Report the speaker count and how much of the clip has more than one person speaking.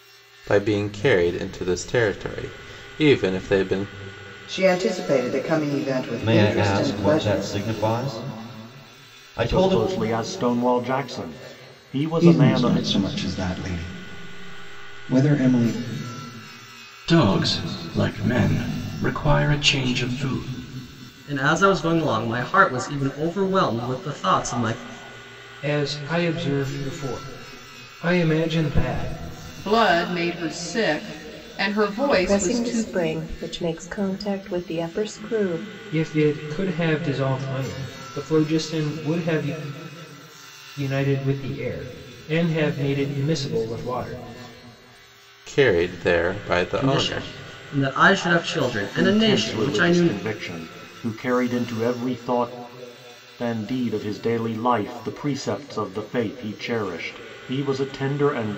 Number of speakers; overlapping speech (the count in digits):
10, about 9%